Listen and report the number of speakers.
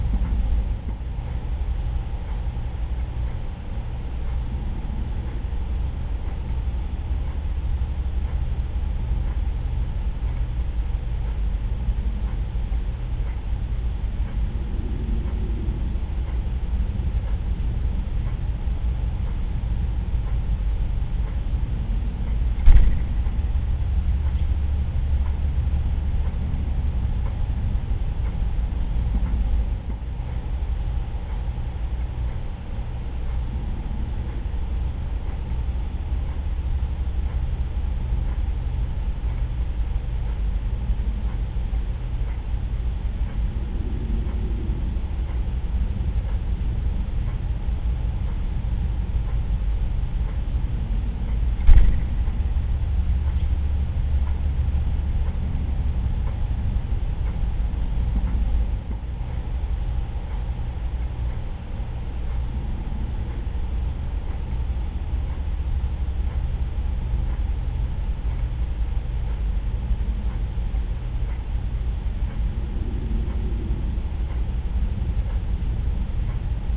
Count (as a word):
zero